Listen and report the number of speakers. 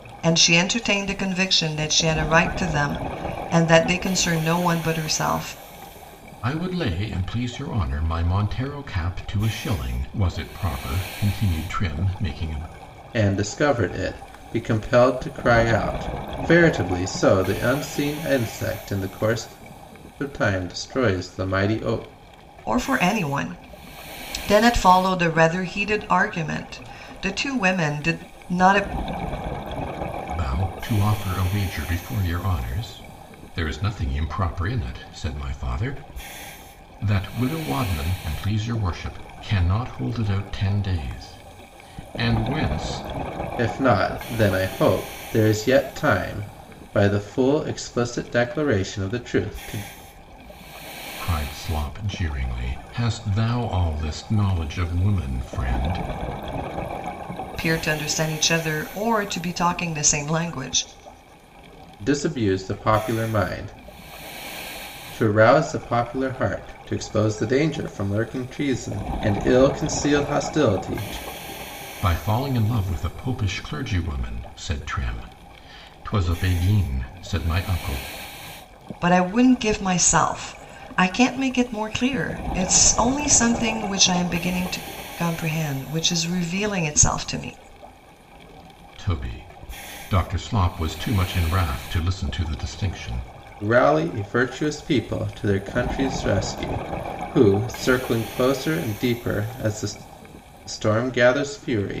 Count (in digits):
3